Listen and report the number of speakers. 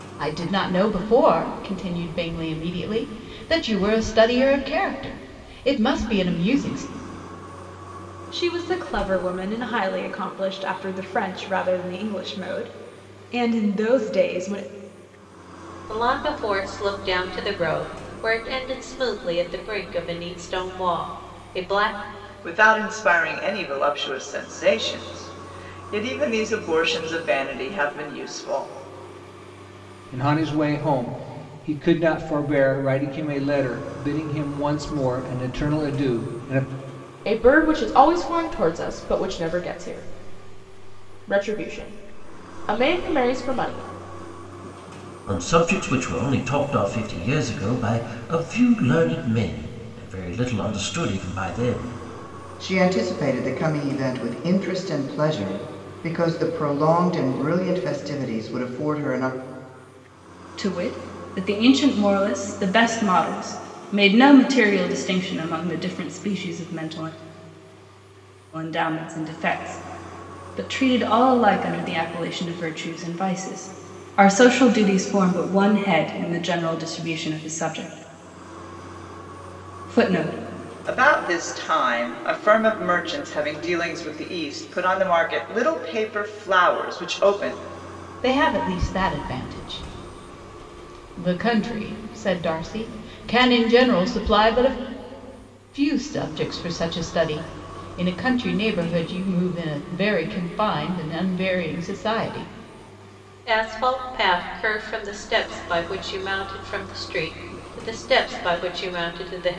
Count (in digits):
9